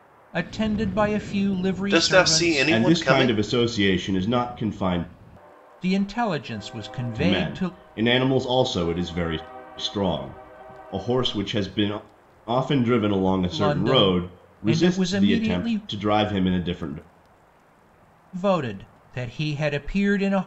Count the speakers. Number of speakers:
three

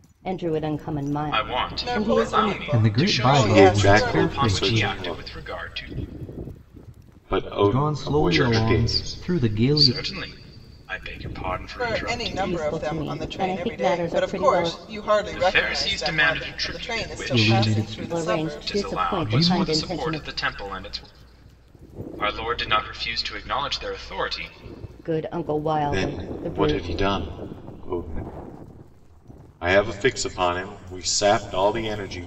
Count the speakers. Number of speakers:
five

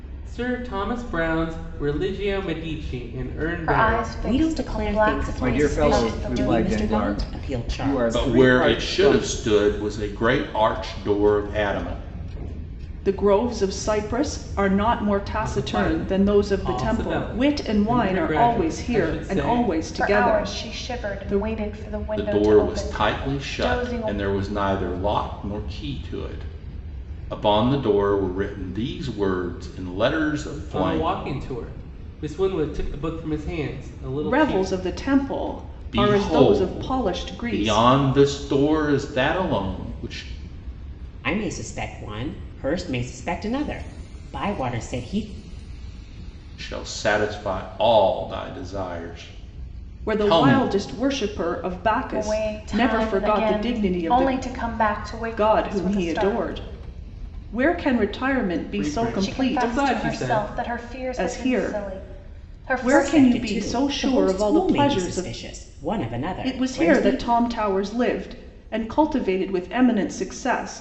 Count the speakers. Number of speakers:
six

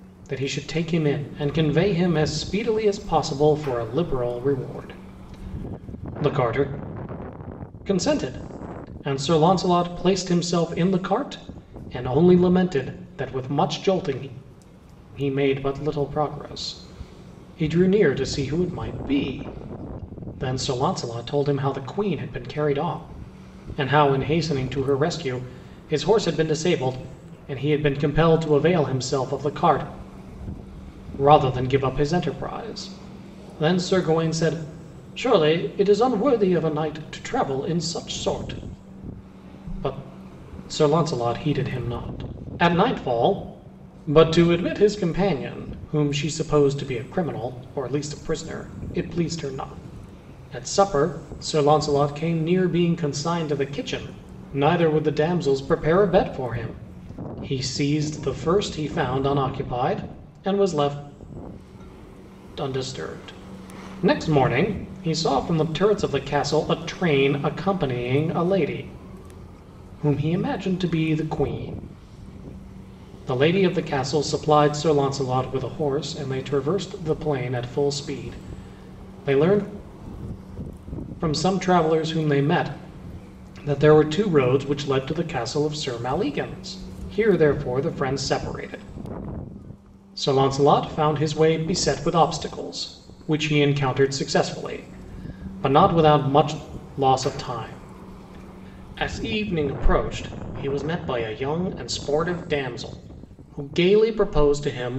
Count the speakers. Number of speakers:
one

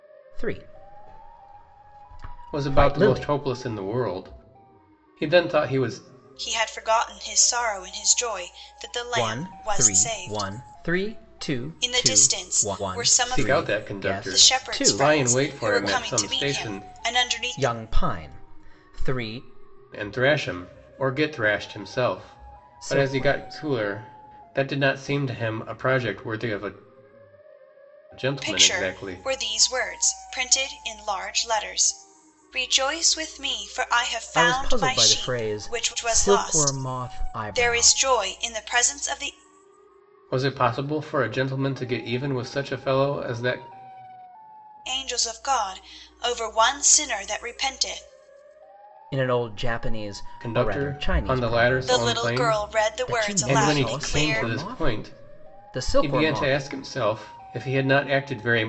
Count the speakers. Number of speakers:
three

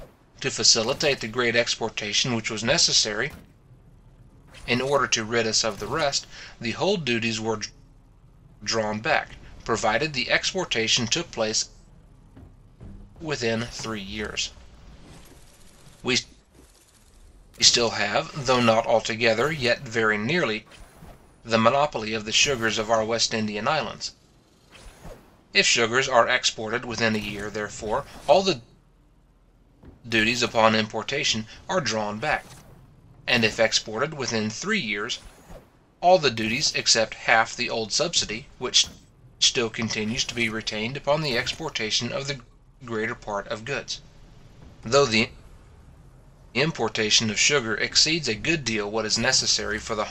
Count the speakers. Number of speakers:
one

